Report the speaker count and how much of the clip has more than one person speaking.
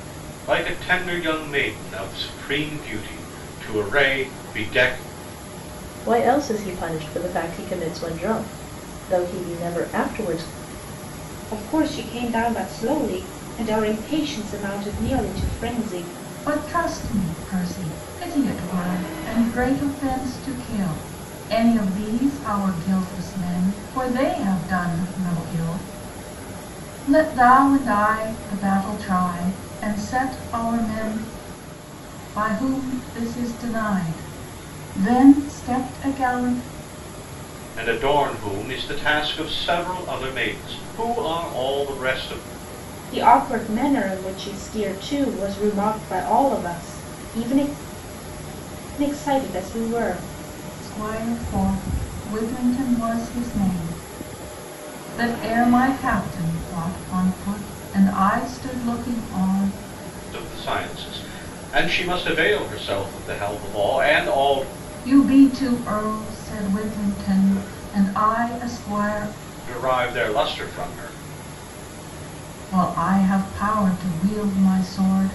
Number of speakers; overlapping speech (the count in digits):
4, no overlap